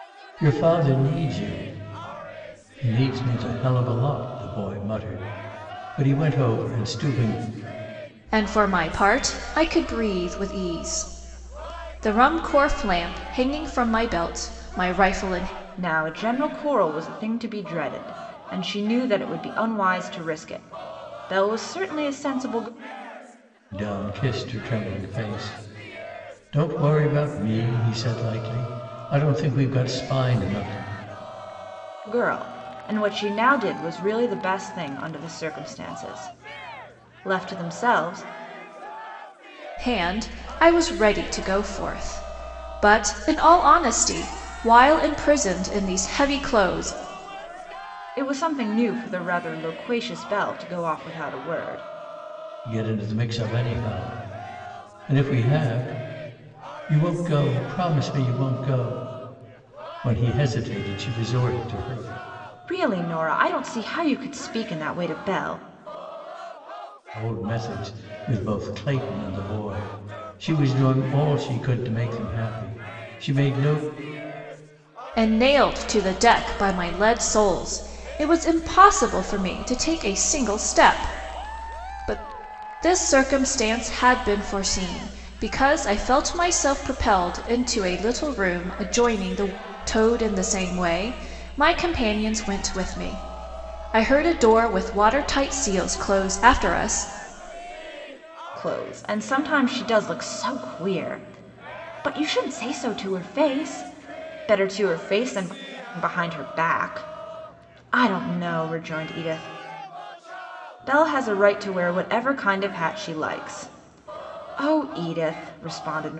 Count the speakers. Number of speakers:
3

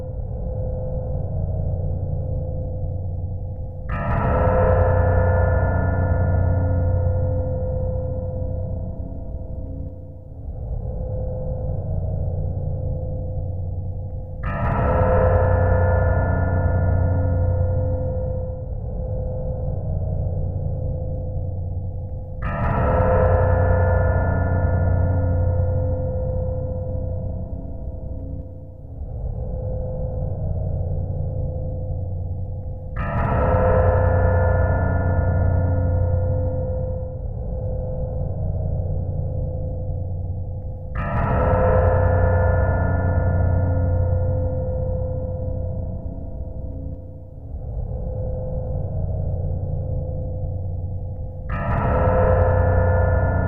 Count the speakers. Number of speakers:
0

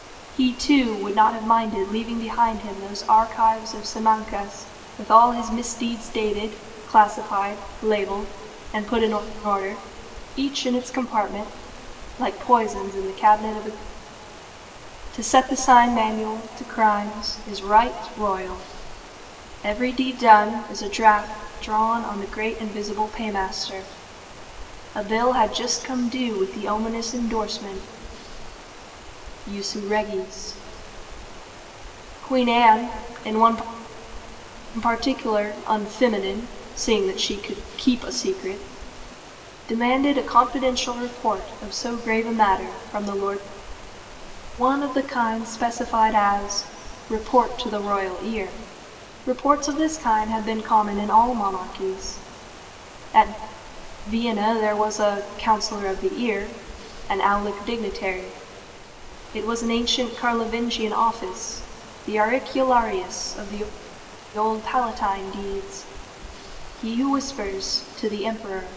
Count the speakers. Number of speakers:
1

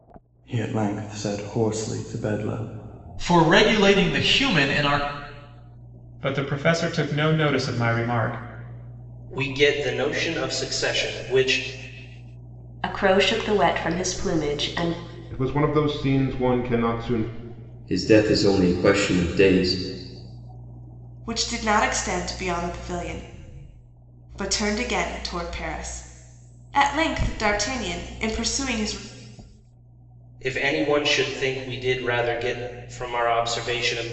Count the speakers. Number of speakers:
8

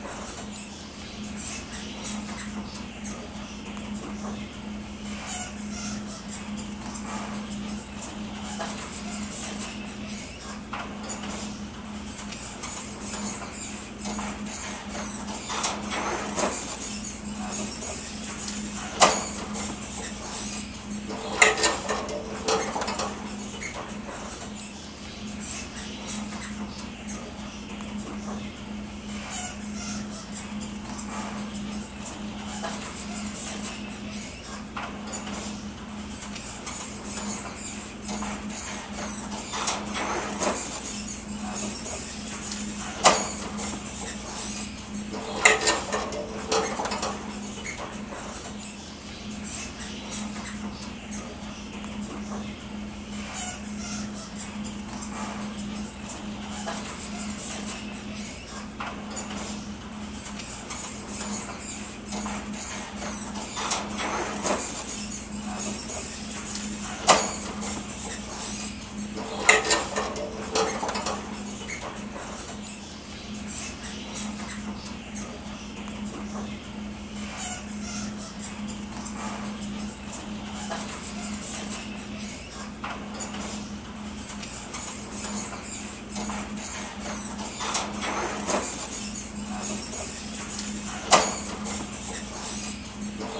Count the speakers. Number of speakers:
0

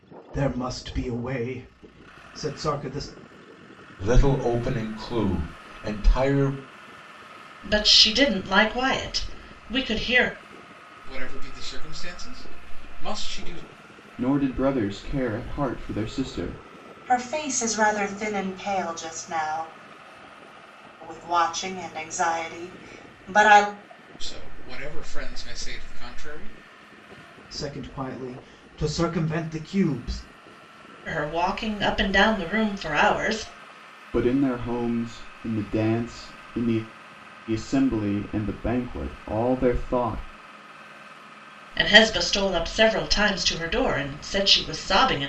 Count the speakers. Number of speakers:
6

